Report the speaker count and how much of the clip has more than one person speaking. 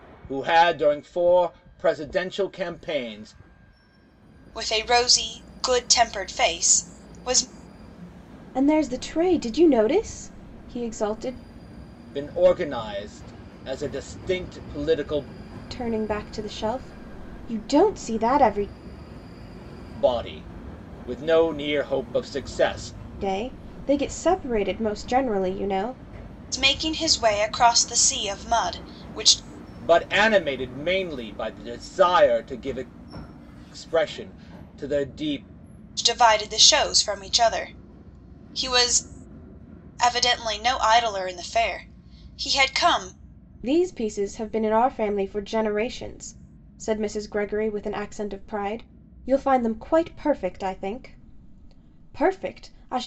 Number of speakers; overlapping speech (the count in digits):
3, no overlap